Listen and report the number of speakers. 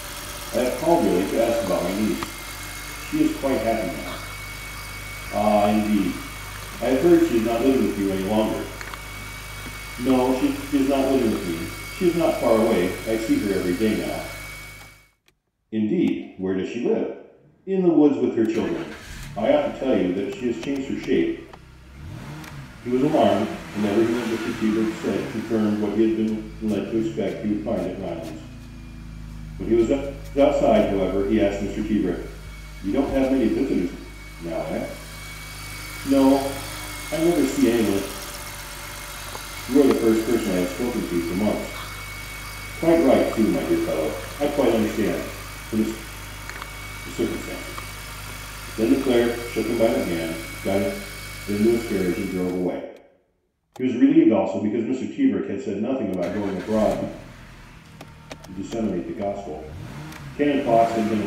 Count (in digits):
1